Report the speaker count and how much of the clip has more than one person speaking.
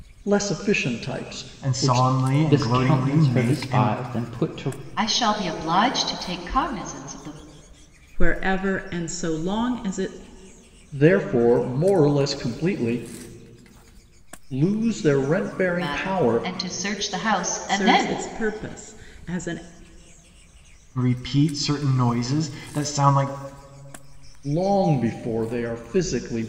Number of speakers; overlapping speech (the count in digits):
5, about 12%